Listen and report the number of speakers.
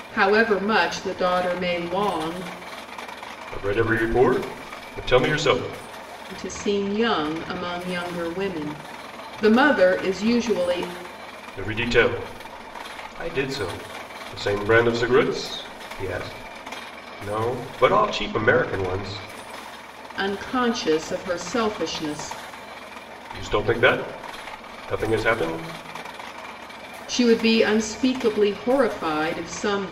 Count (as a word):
two